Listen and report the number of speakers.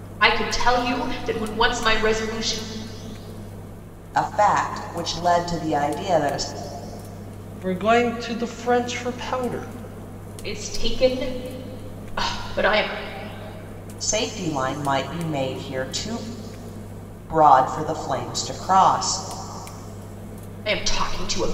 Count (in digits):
3